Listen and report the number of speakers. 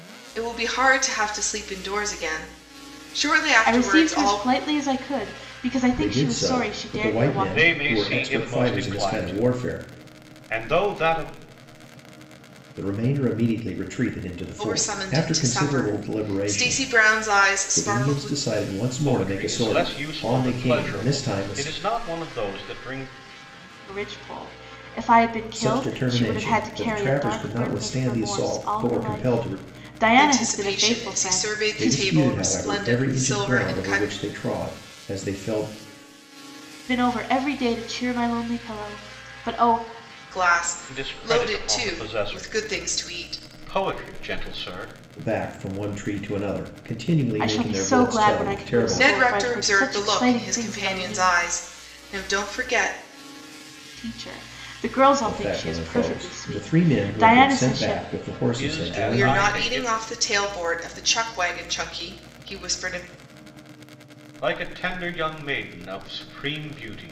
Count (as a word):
four